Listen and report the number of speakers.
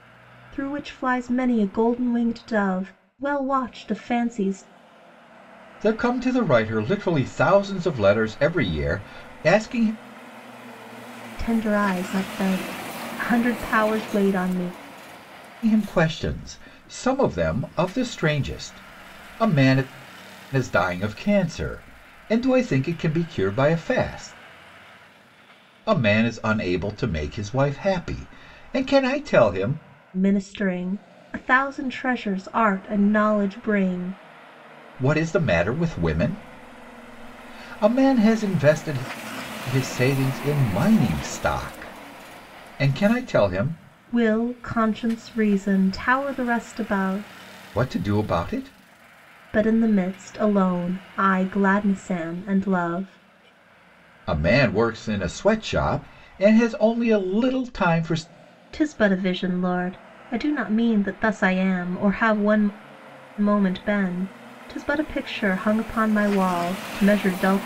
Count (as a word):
two